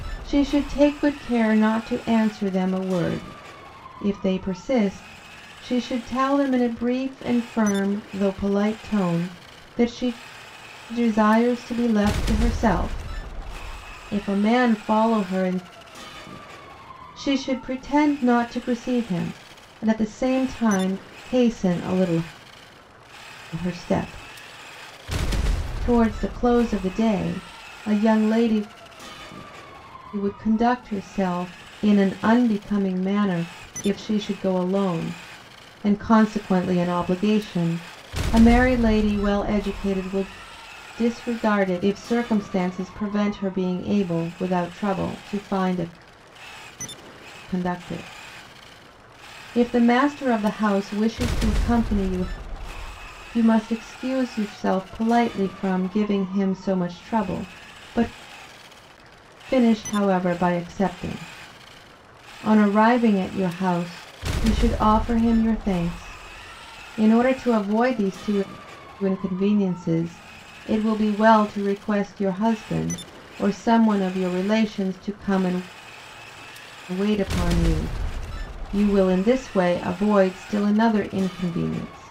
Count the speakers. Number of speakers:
1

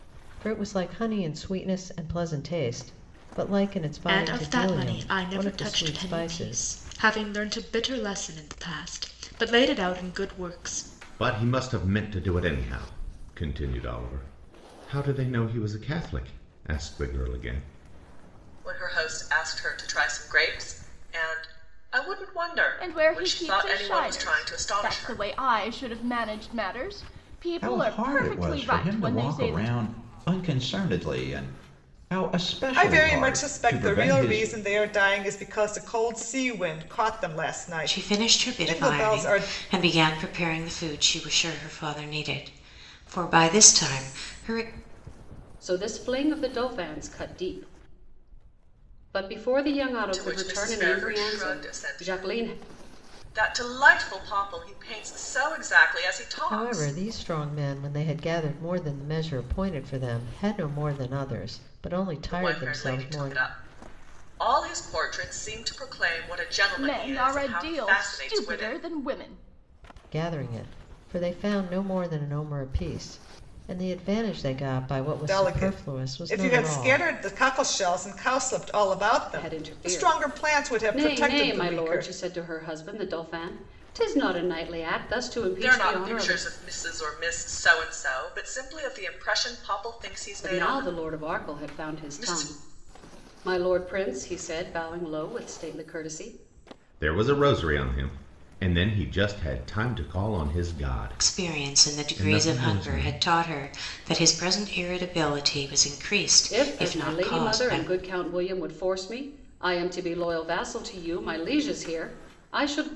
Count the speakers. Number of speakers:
9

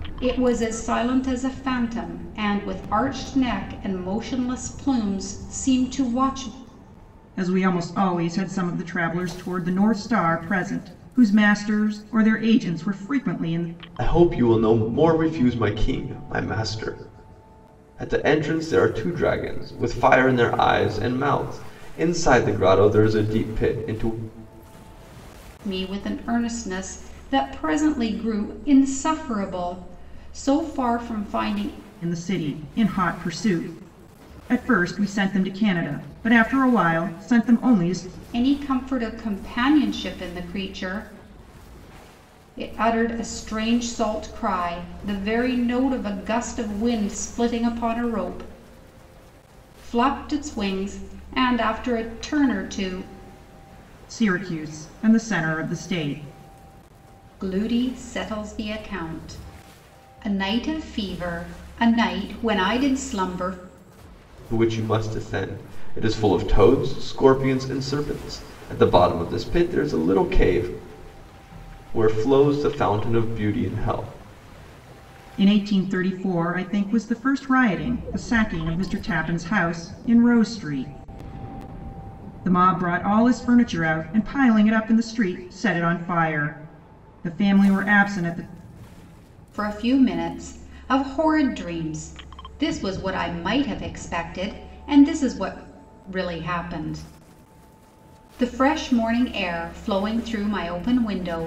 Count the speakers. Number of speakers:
3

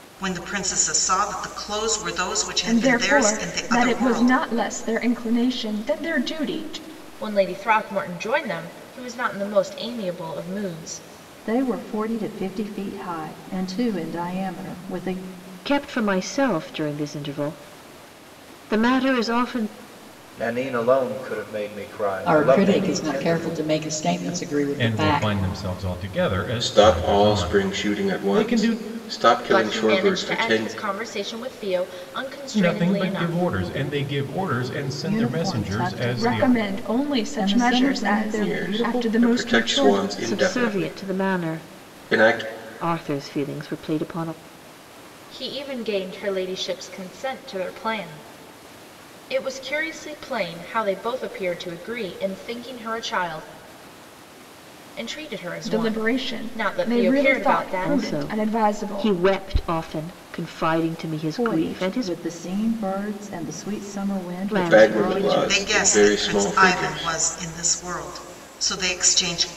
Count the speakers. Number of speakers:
9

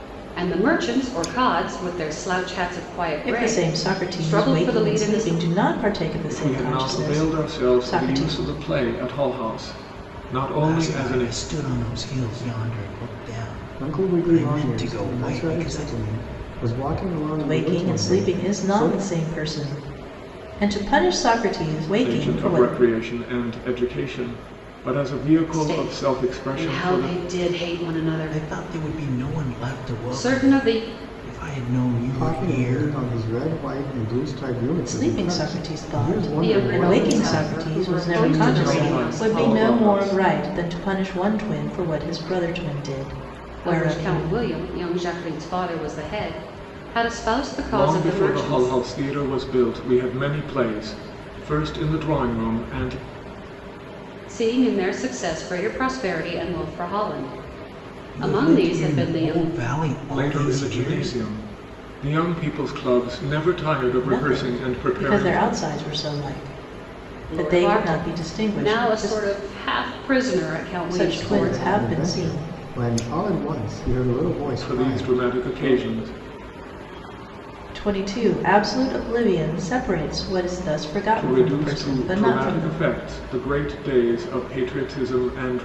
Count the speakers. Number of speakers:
5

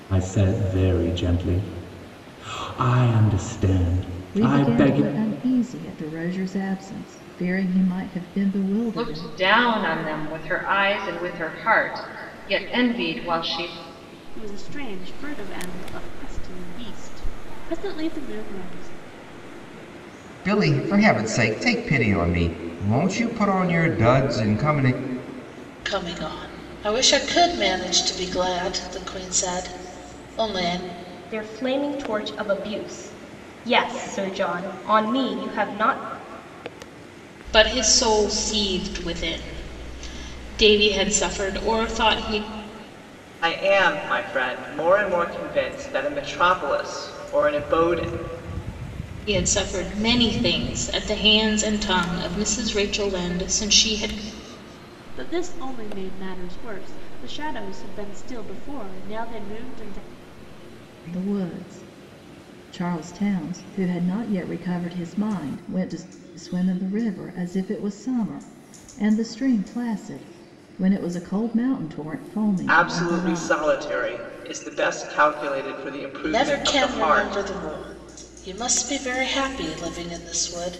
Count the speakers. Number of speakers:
9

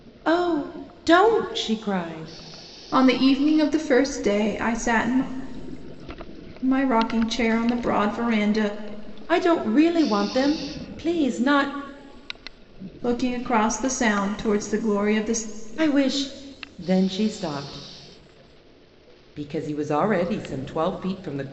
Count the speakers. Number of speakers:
2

